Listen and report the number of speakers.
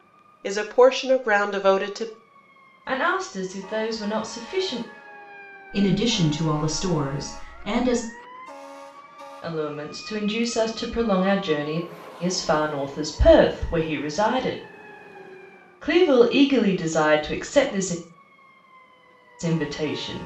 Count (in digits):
3